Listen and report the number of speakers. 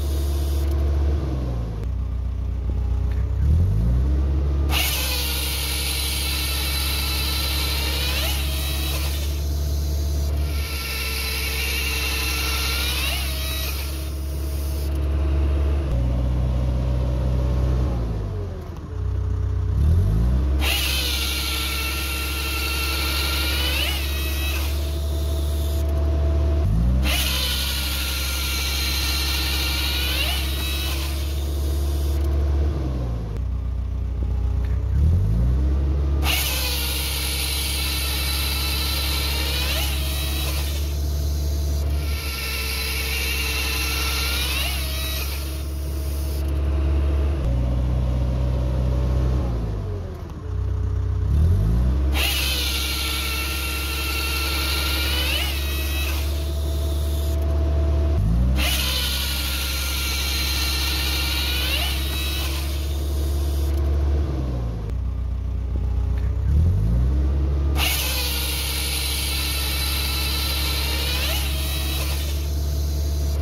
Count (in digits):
0